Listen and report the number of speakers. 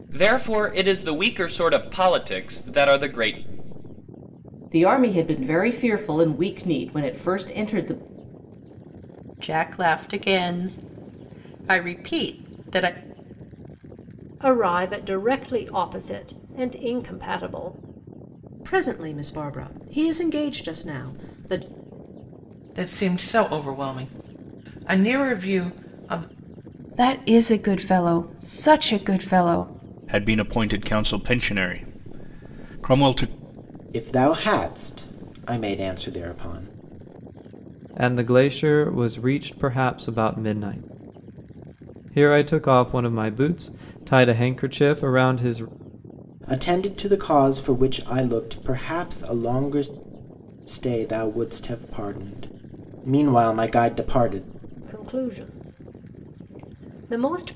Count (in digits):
10